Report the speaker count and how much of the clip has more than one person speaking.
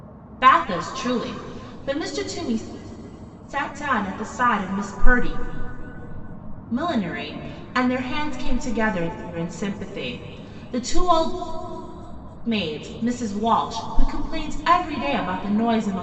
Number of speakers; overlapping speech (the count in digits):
1, no overlap